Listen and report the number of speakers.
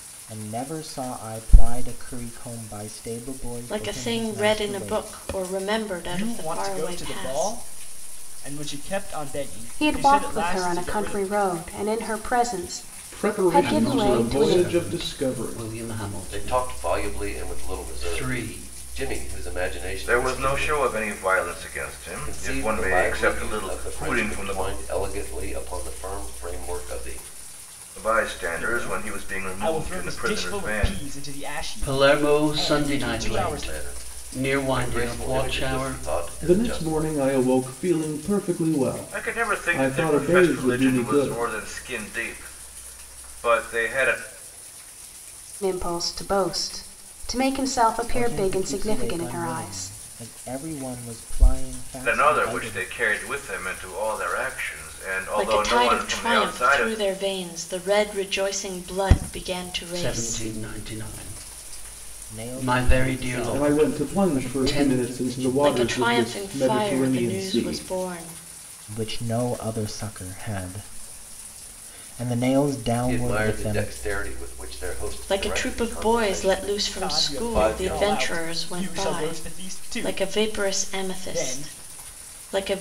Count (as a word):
eight